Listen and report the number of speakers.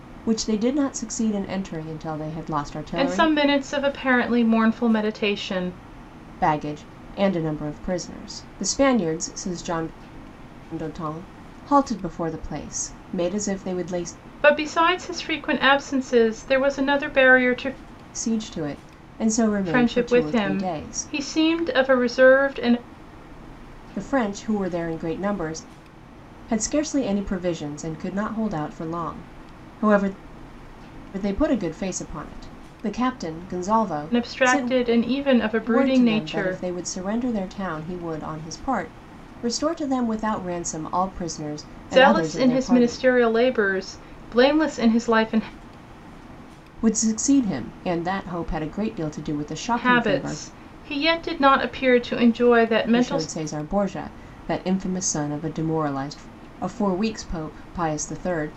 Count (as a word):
two